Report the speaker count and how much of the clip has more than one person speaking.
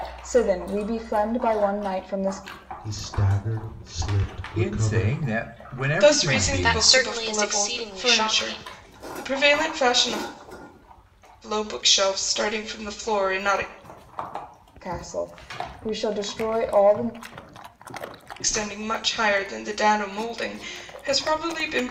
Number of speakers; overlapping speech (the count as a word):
five, about 15%